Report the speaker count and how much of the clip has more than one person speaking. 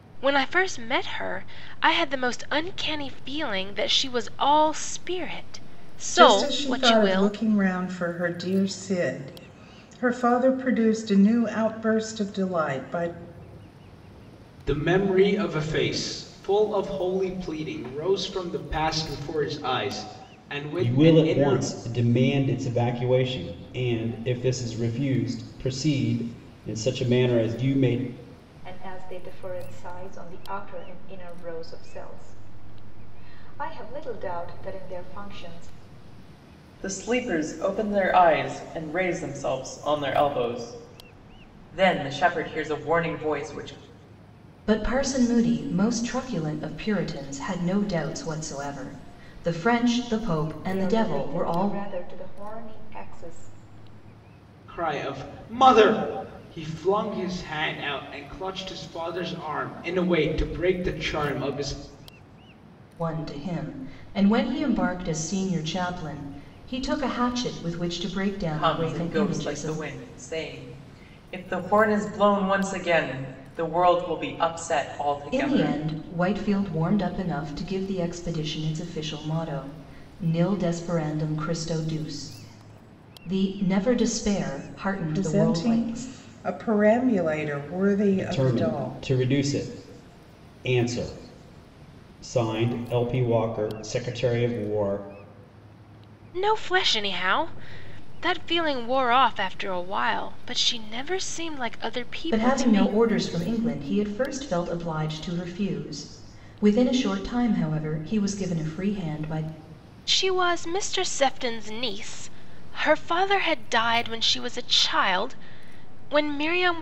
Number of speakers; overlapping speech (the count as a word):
seven, about 7%